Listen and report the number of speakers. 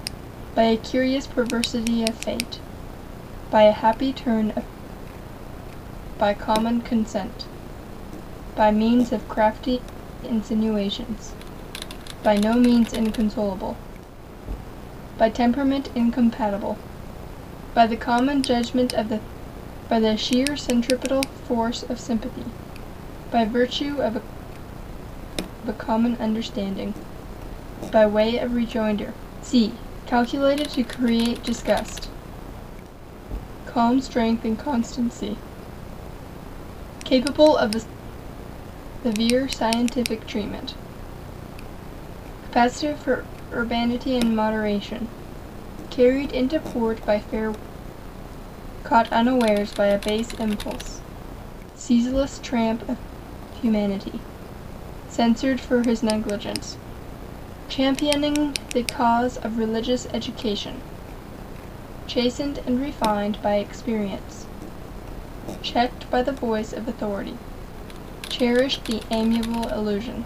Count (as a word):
one